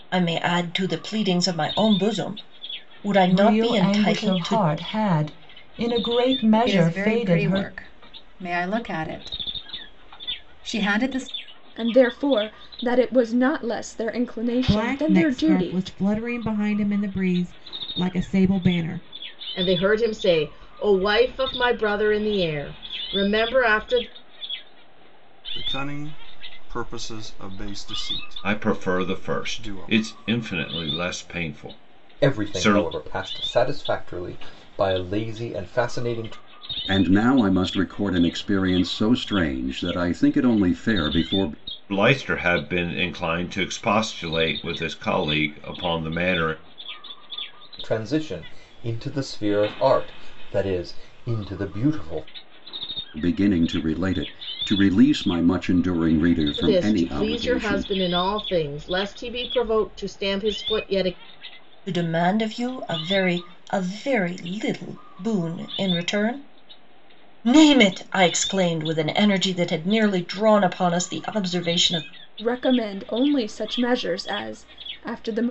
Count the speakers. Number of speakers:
10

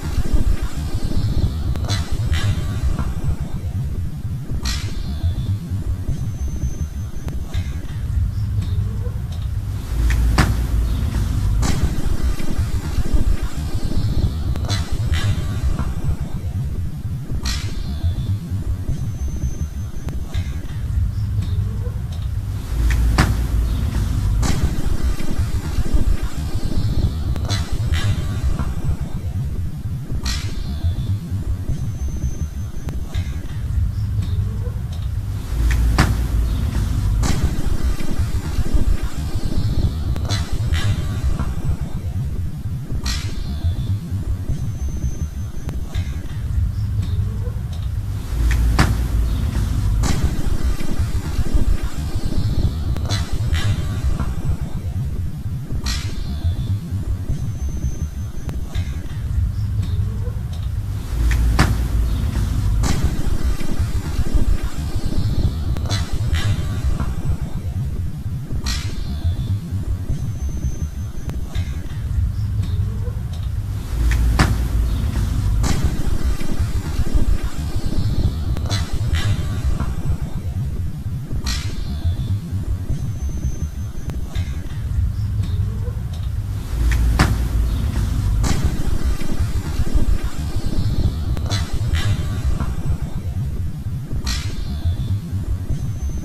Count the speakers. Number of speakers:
0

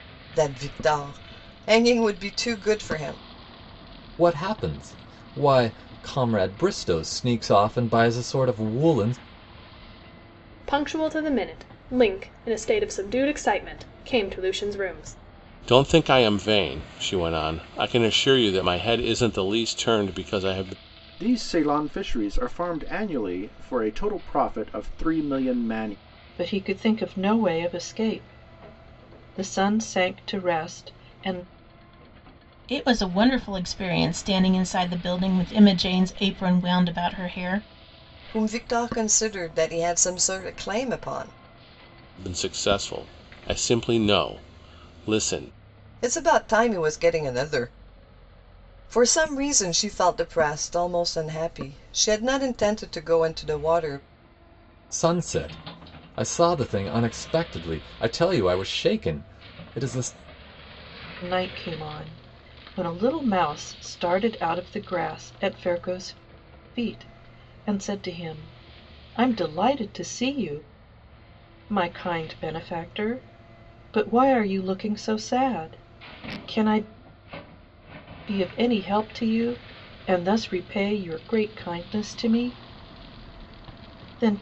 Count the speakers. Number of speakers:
7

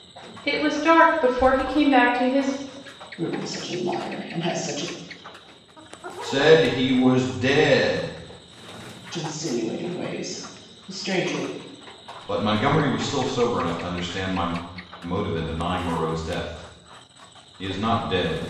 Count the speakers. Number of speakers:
3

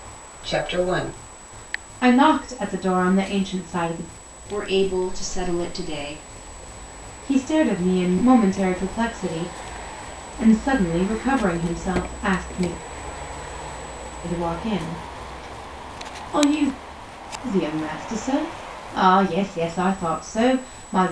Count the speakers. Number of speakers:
3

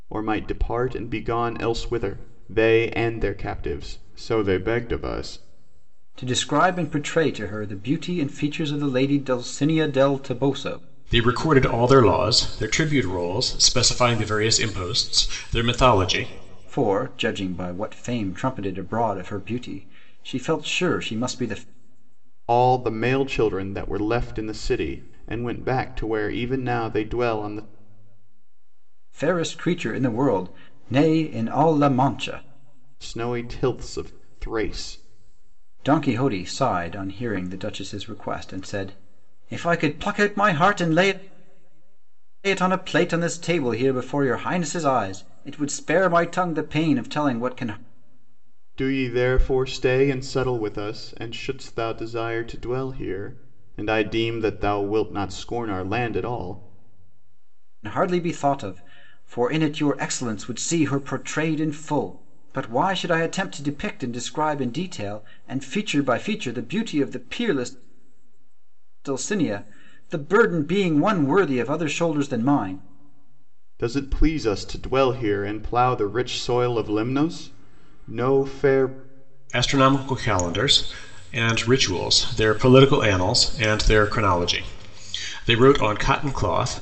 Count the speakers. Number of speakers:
3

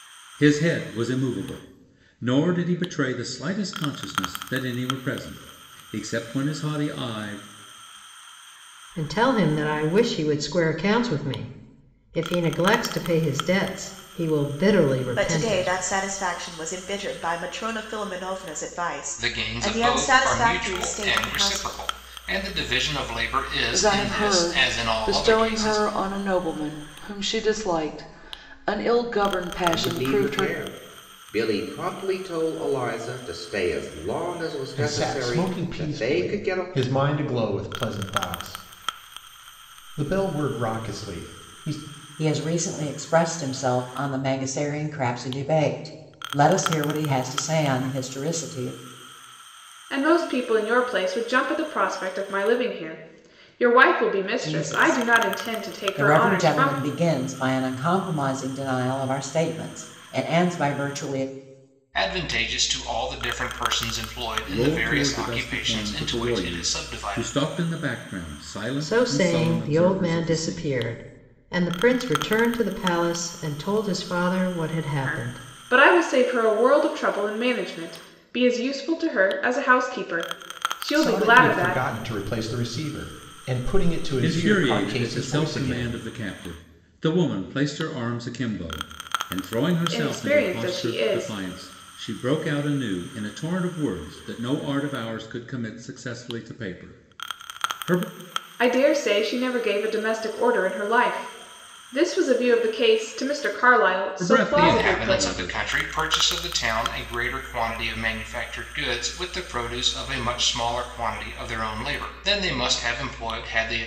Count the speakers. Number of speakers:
9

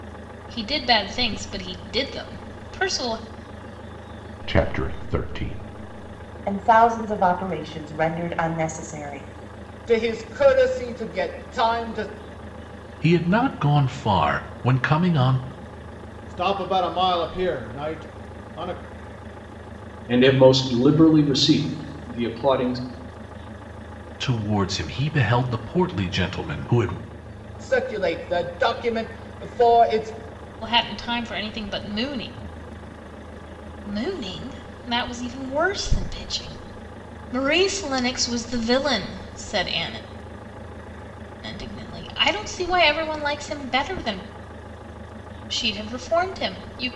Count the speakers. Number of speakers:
7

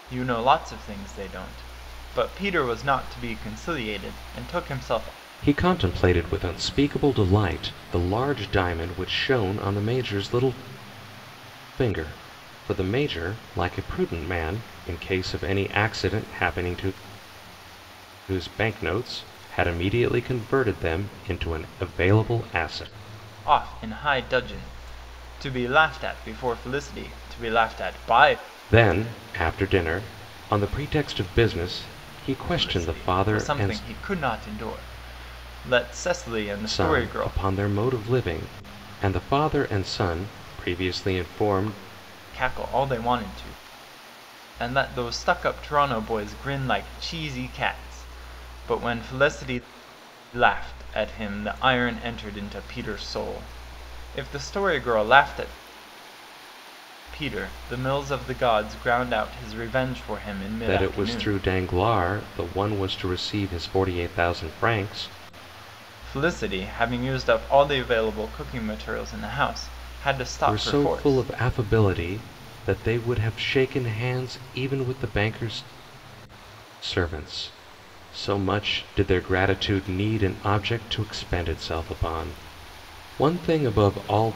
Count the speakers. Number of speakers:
2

